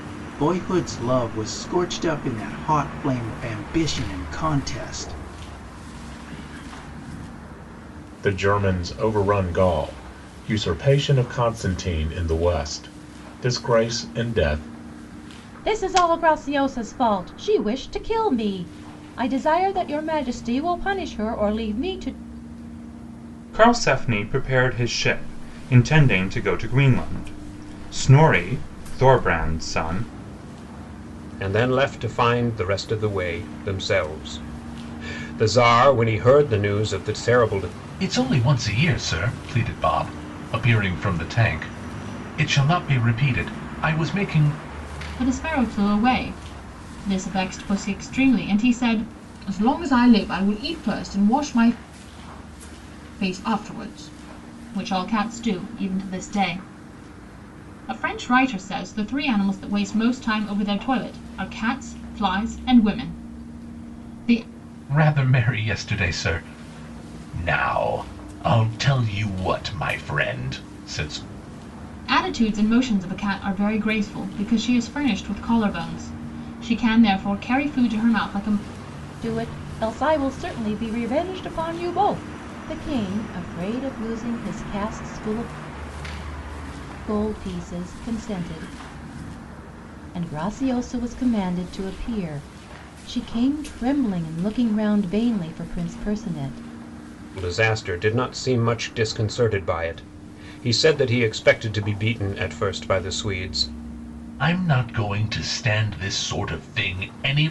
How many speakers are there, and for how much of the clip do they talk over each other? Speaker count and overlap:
7, no overlap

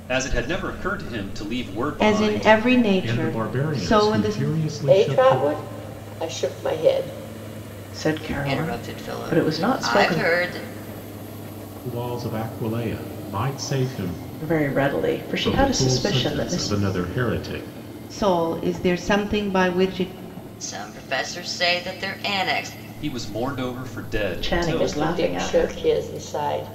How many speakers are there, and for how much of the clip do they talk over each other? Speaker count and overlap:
6, about 27%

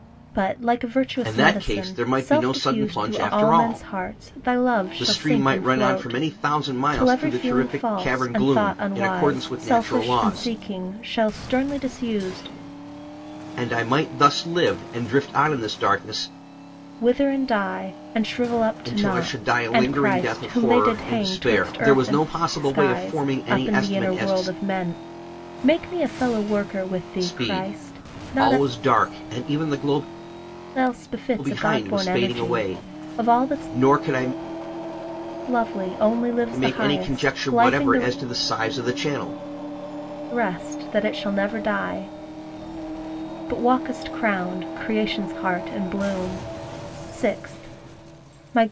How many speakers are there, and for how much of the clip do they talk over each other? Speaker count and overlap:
2, about 37%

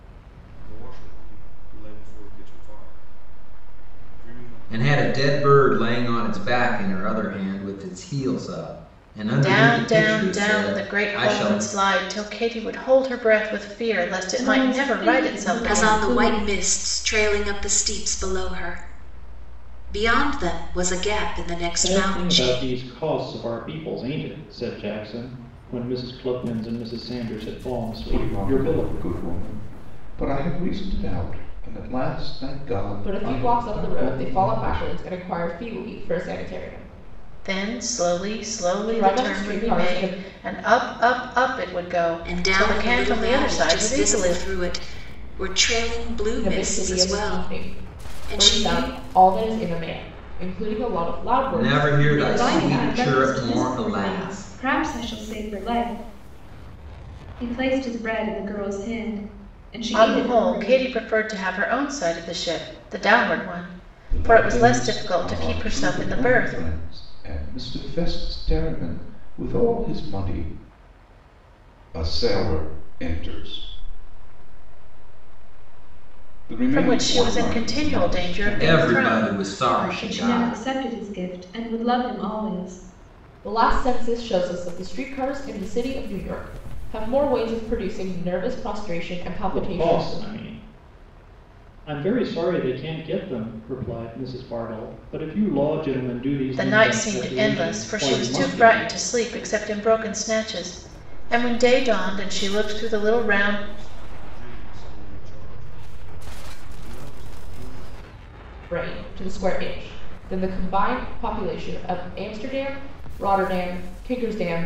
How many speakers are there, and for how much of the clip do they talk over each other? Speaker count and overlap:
8, about 30%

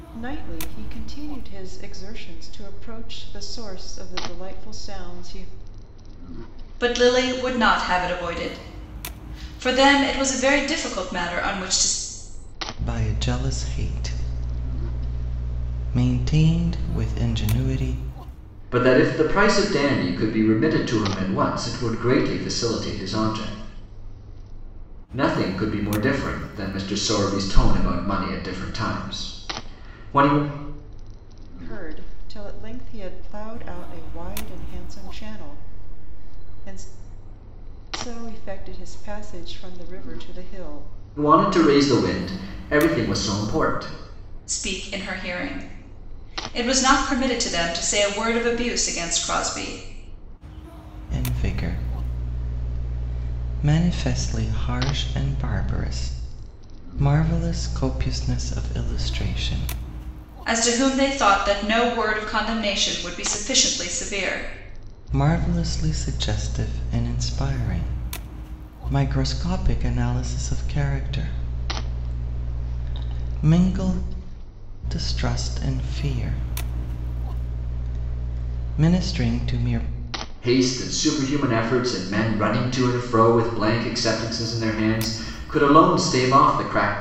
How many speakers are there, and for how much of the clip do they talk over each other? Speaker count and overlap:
4, no overlap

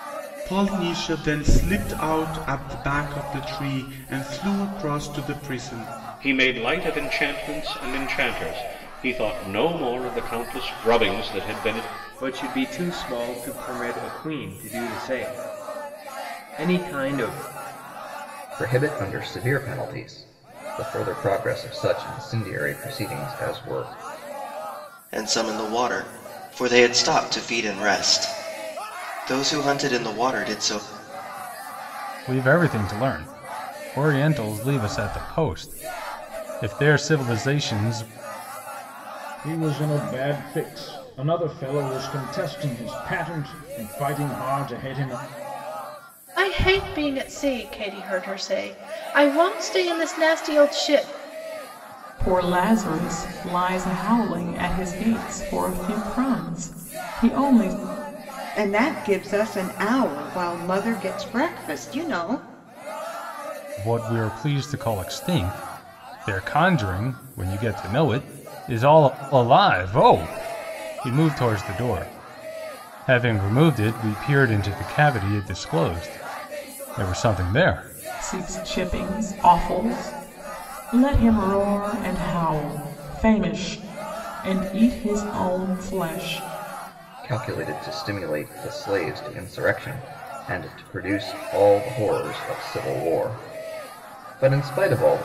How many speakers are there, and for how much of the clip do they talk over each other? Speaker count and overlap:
10, no overlap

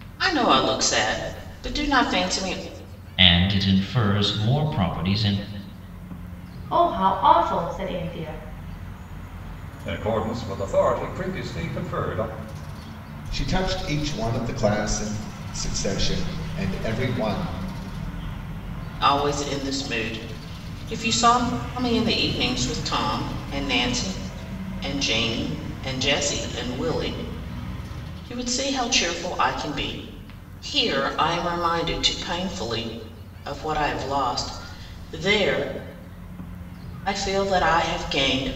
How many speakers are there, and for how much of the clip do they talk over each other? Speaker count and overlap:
5, no overlap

